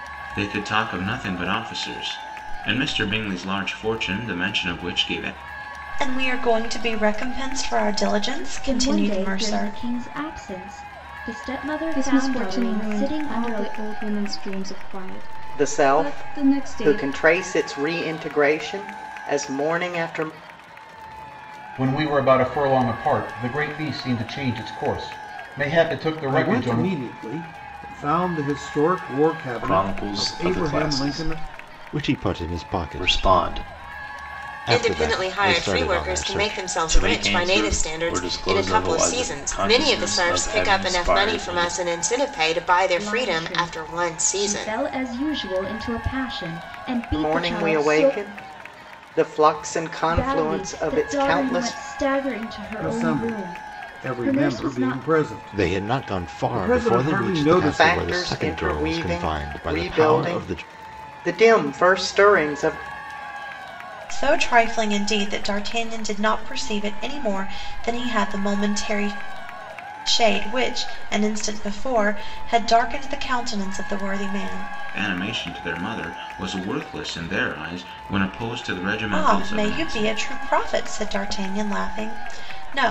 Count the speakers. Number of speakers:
ten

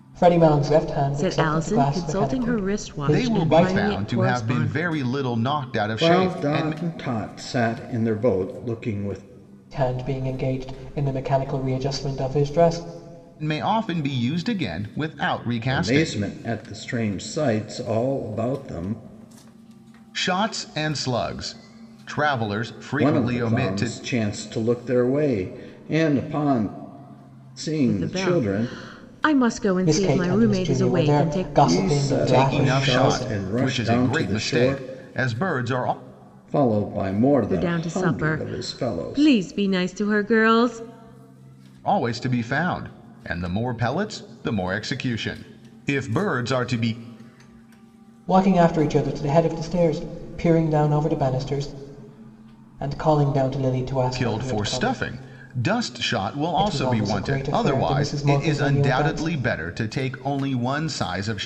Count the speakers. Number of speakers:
four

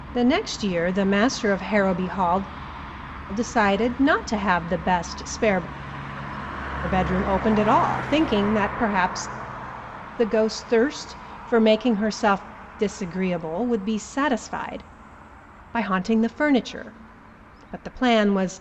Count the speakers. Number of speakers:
one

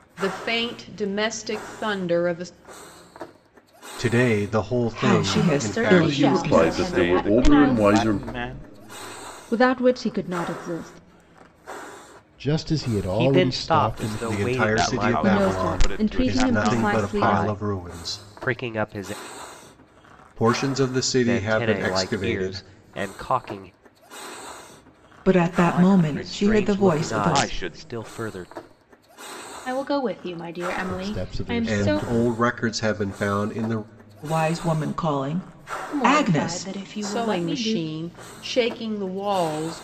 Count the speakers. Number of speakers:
nine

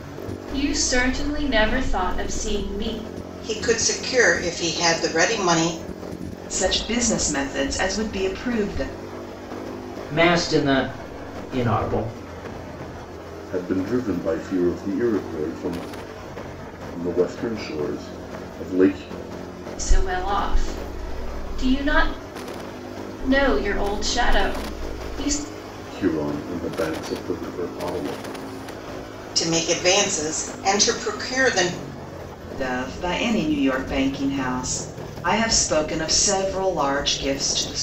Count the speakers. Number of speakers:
five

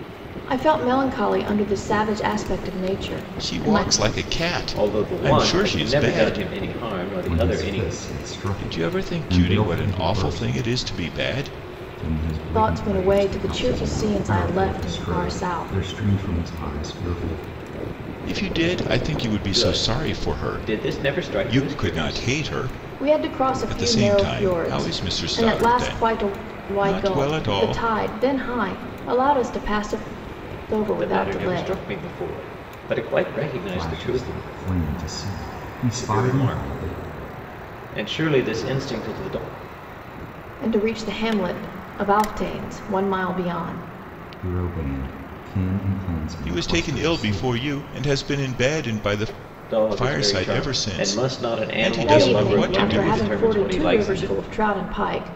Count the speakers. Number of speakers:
four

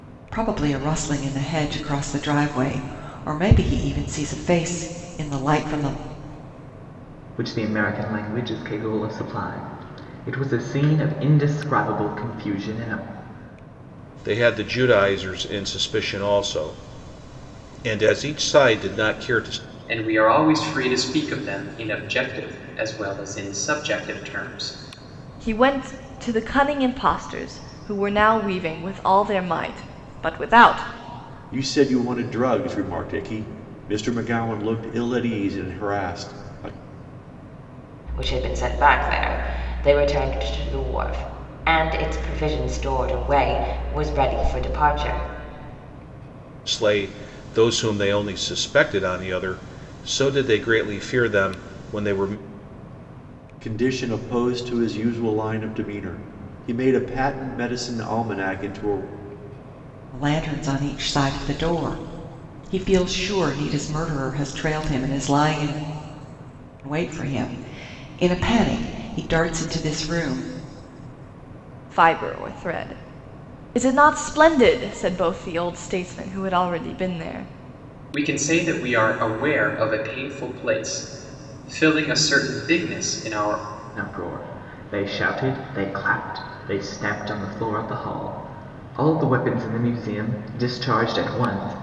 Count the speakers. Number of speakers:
seven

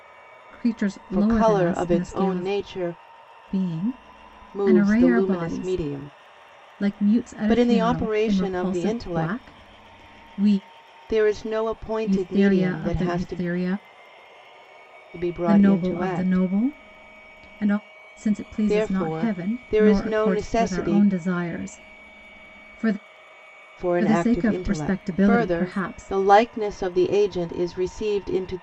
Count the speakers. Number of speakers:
two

